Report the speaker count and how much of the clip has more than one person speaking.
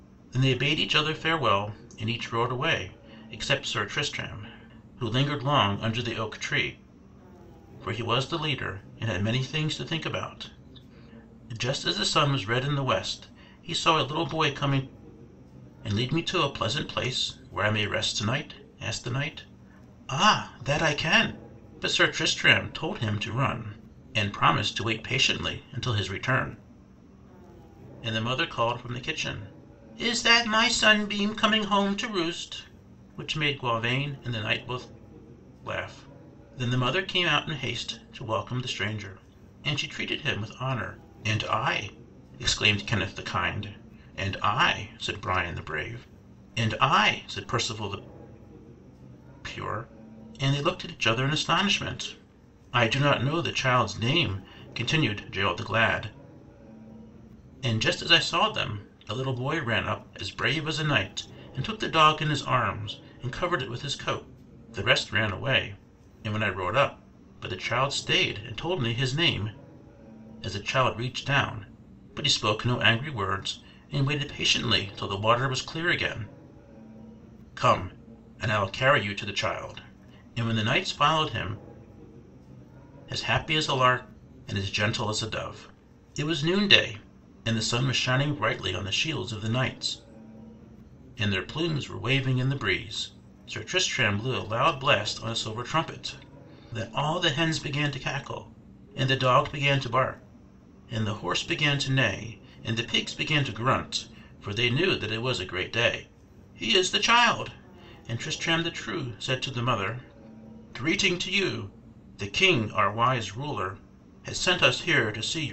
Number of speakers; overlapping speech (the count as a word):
one, no overlap